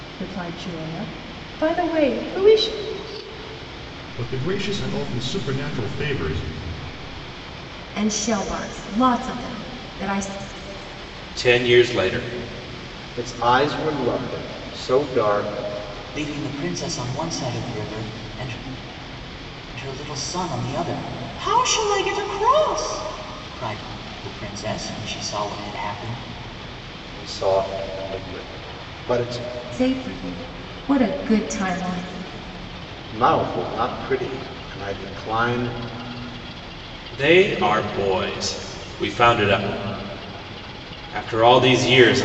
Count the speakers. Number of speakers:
6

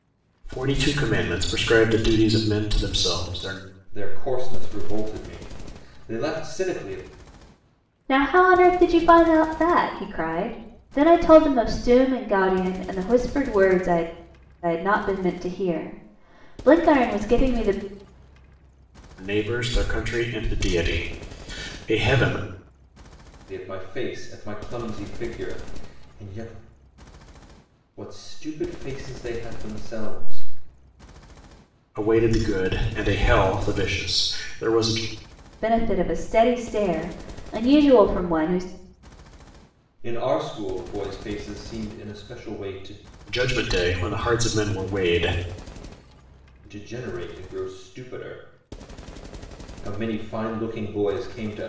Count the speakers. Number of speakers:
3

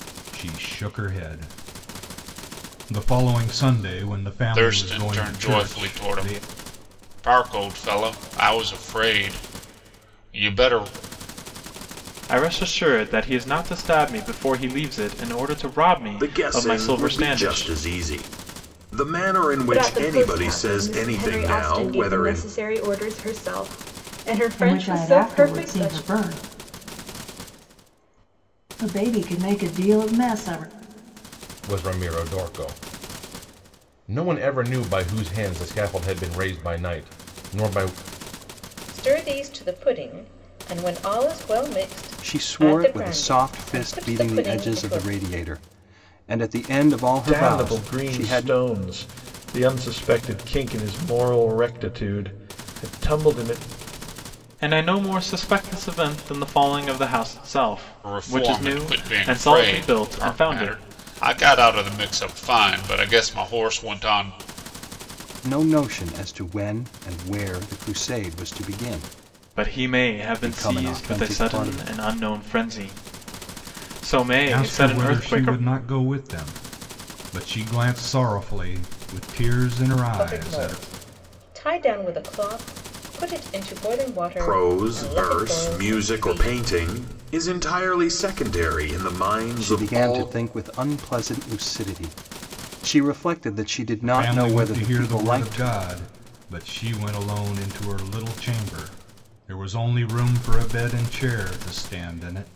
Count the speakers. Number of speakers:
10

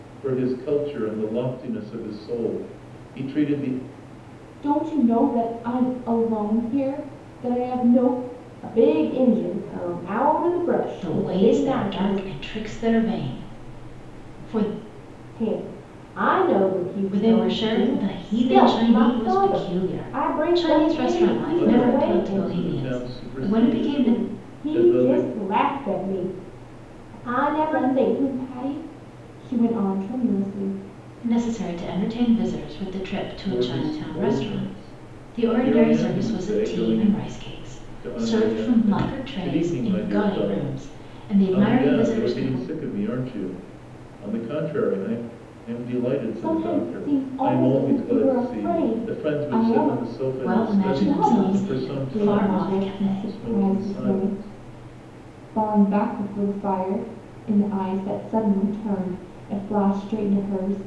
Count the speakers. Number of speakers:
4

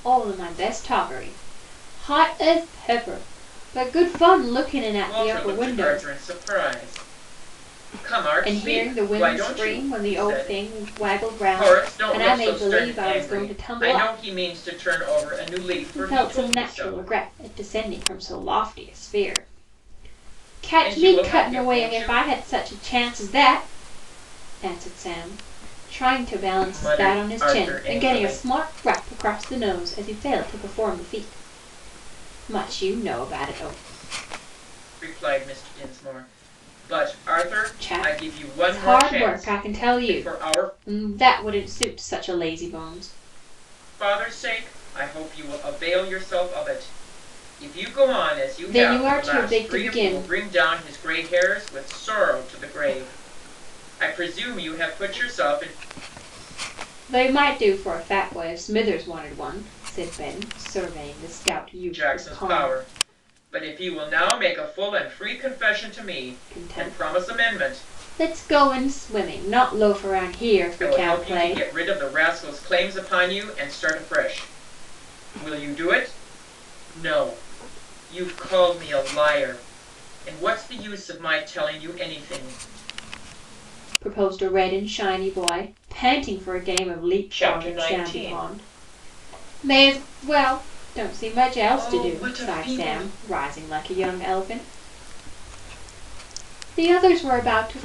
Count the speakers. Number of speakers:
2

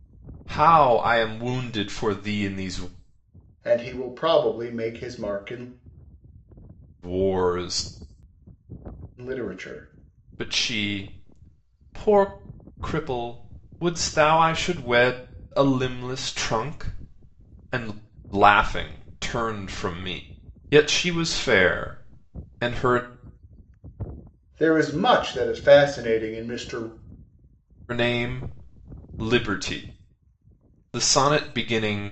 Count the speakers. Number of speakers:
2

